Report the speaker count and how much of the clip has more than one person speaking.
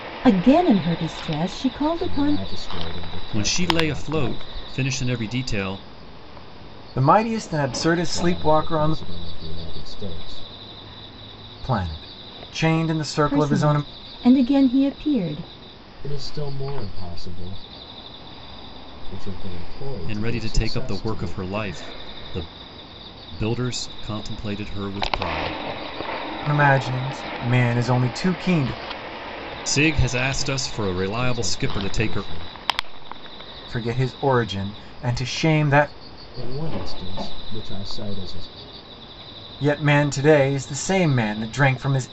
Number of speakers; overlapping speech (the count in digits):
4, about 14%